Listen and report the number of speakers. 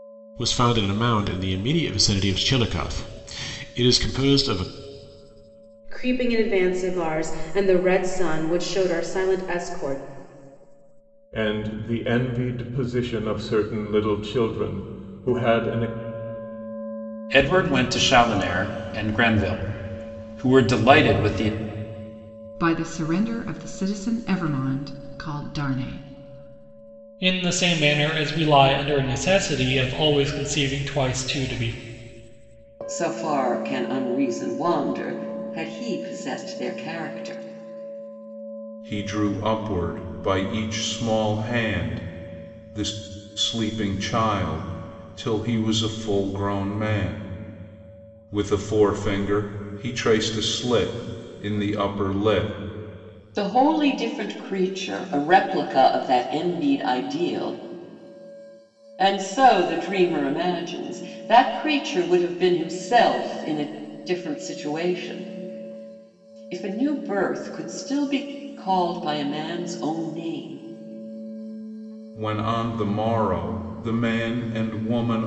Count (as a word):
eight